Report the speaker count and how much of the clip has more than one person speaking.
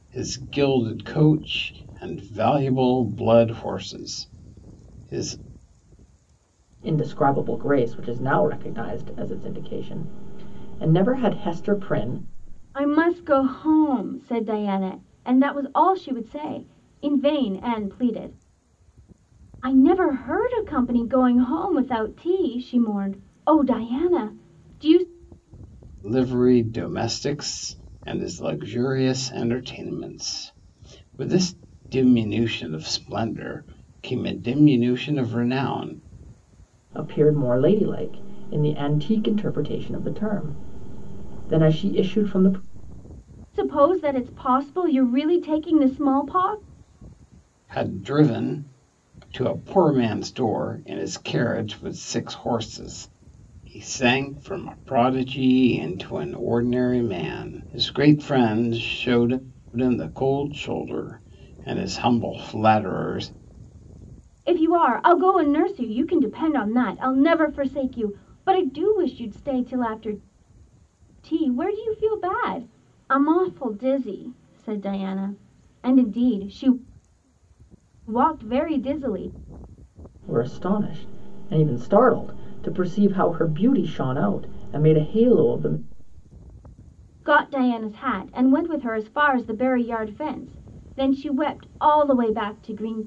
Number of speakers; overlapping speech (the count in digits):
3, no overlap